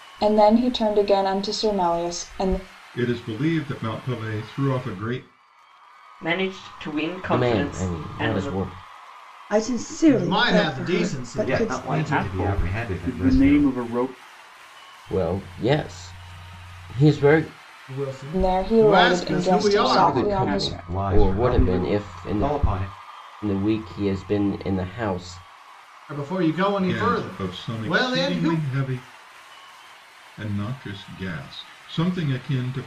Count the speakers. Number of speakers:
8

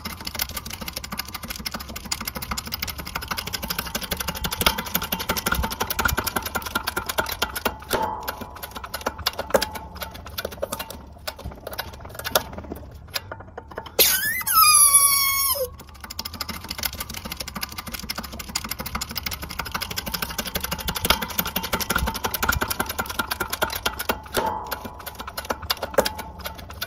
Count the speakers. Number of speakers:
0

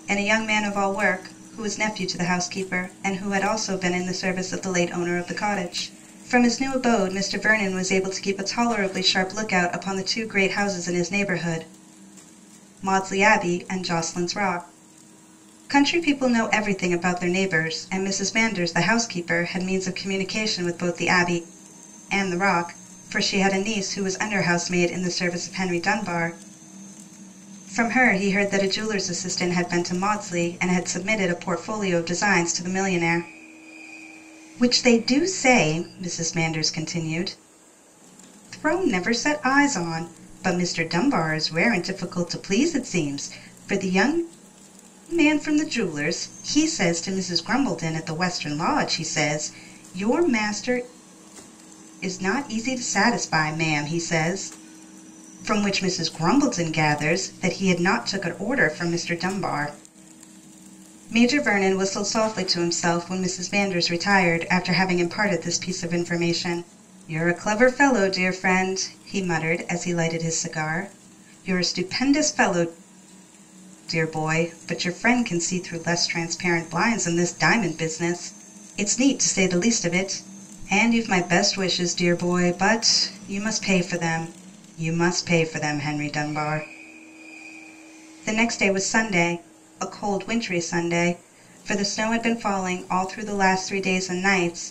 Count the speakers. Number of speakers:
1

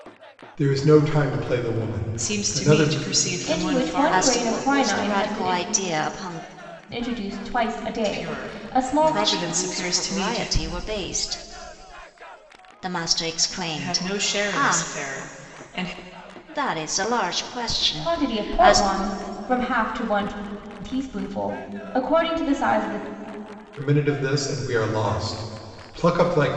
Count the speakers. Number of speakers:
4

